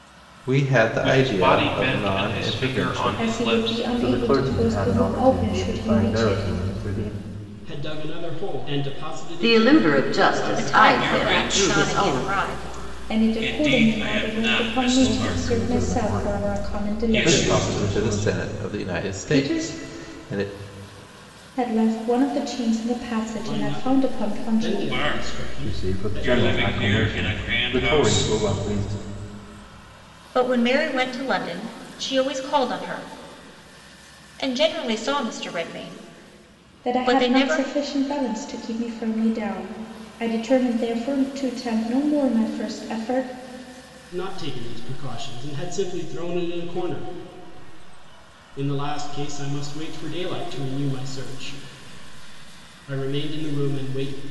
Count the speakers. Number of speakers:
eight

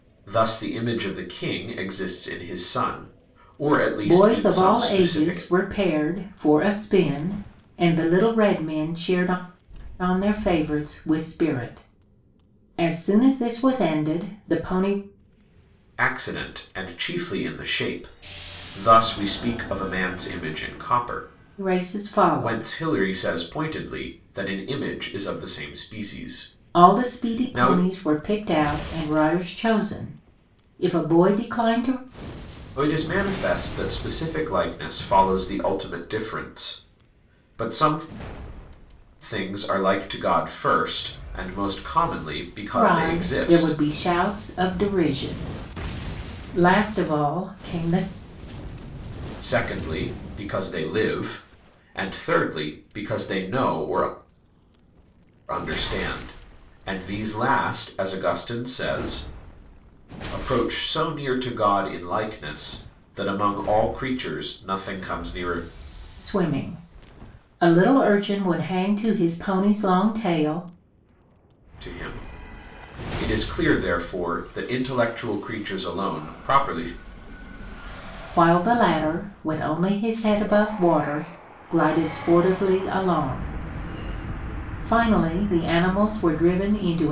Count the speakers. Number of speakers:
two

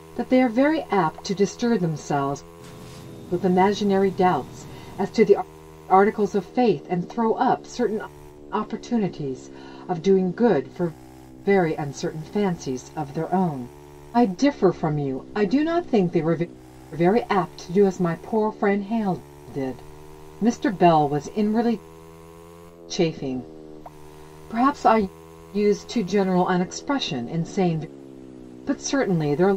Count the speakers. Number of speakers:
one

